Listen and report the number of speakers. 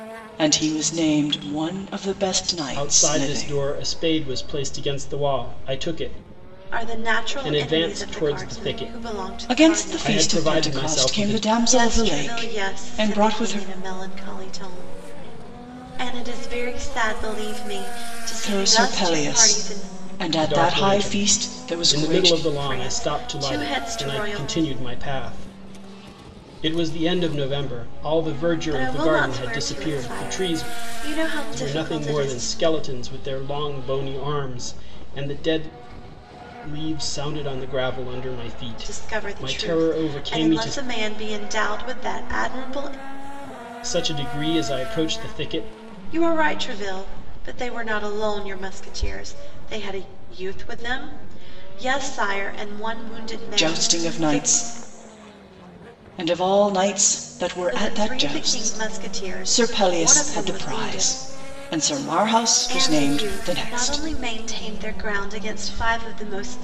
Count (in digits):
3